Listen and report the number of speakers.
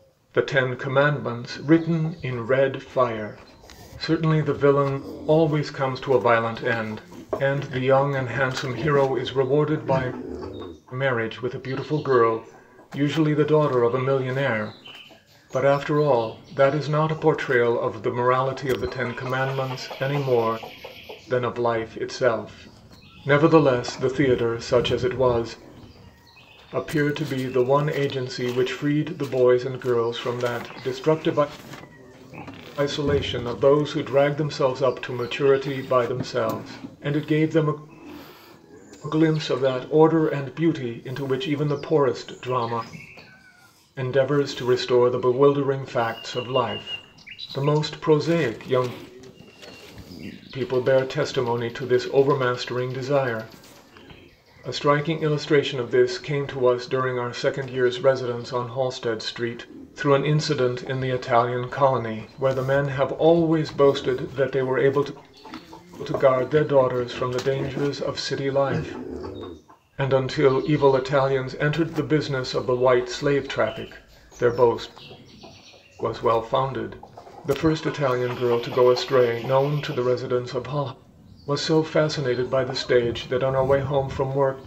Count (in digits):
1